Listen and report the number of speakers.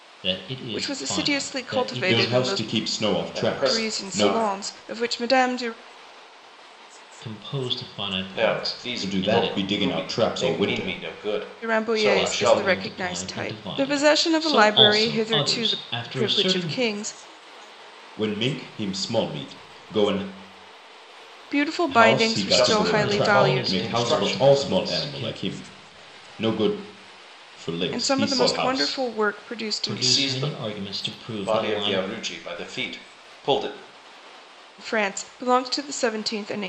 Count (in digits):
4